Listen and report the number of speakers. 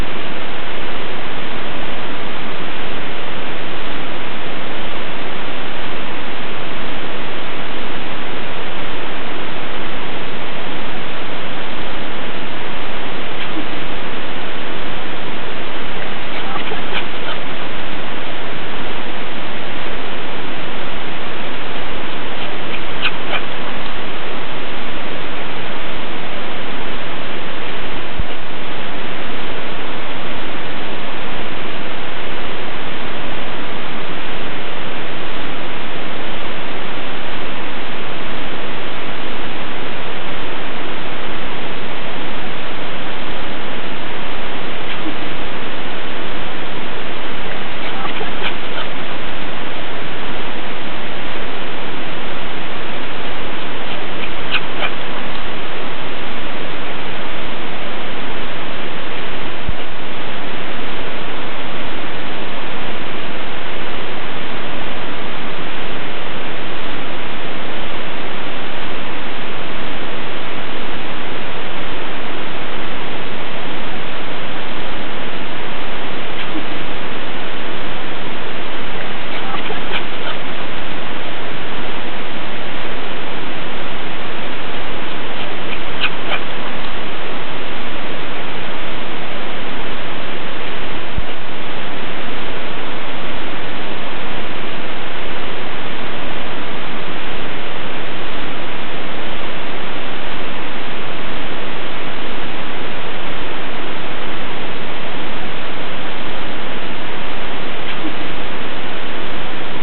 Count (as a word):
zero